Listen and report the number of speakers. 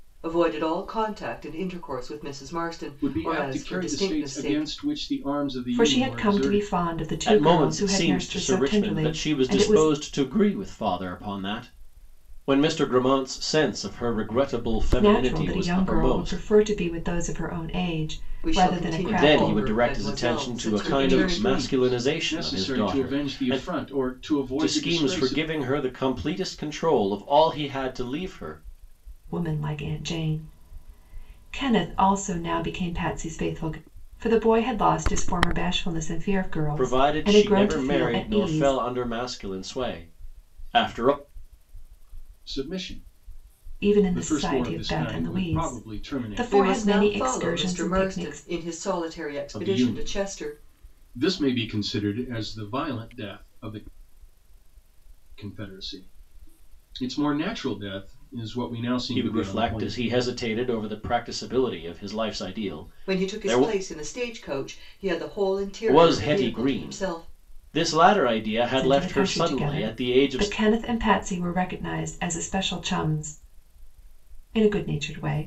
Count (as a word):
four